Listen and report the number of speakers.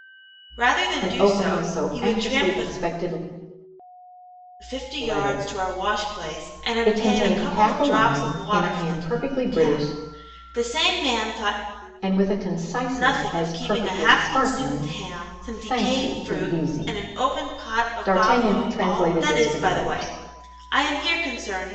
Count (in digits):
2